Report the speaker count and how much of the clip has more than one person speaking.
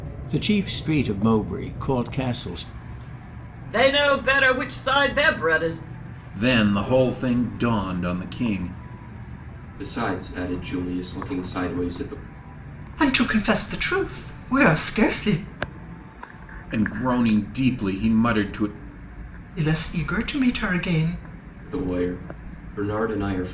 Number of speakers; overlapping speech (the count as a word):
five, no overlap